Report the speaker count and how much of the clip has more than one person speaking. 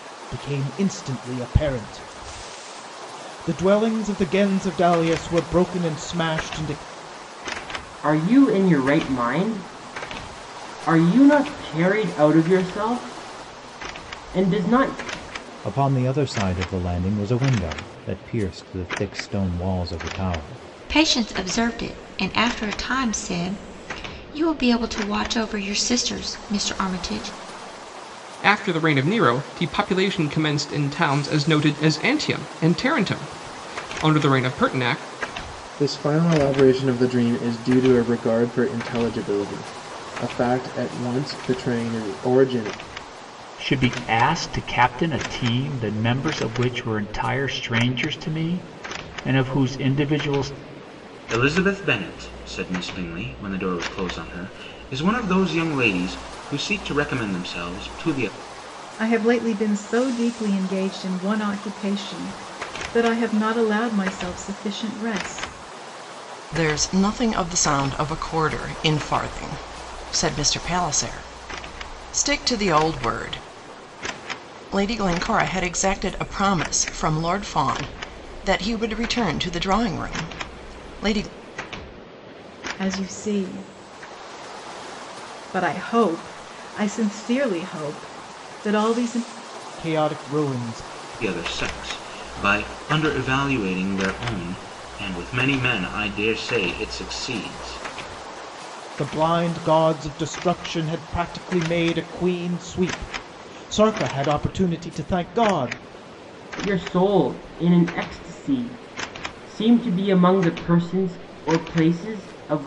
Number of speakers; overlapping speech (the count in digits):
10, no overlap